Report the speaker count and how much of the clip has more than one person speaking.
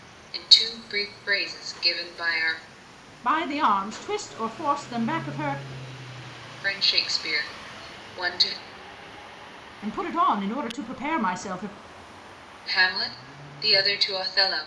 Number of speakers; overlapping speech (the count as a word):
two, no overlap